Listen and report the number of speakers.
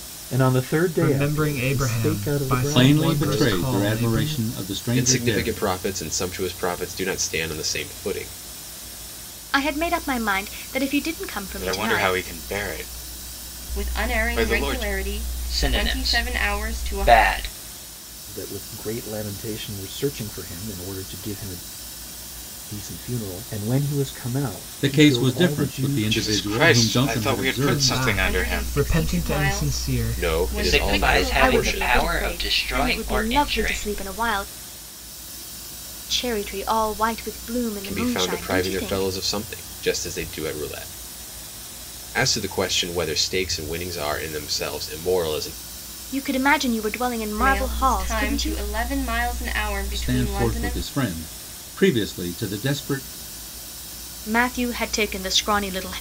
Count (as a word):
eight